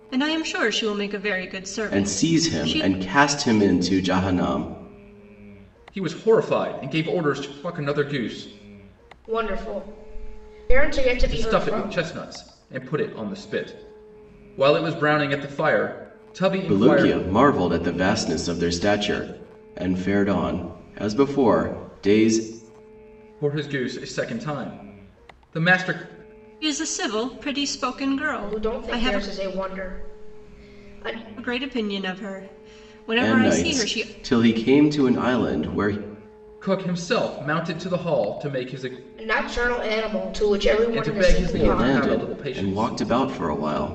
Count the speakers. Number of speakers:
four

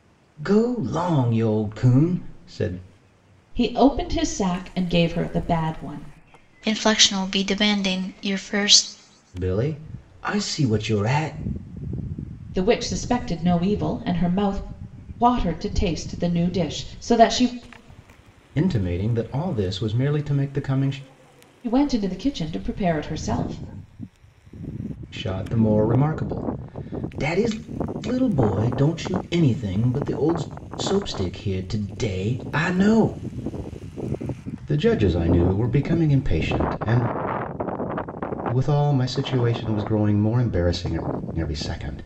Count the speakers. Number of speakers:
three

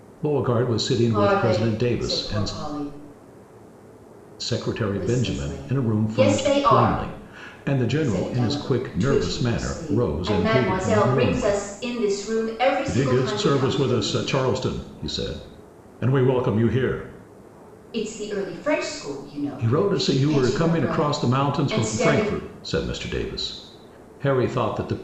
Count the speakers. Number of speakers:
two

